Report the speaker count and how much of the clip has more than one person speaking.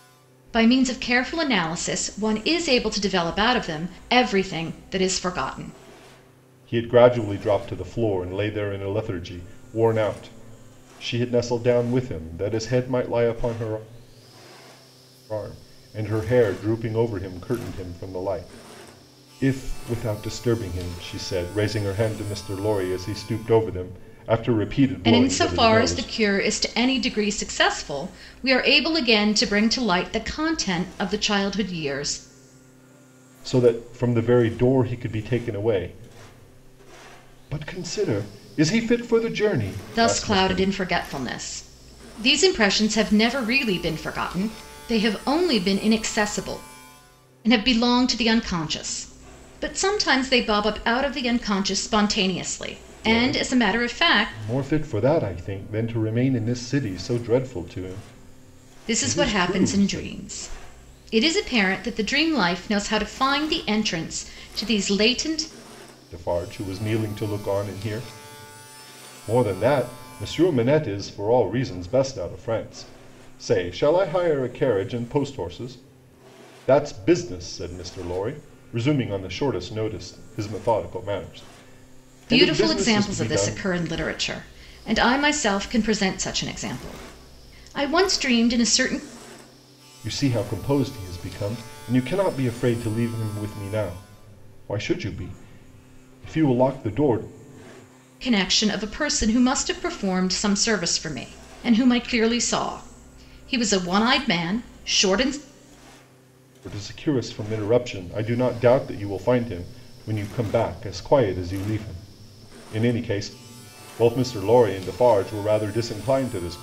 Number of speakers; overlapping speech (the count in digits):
2, about 5%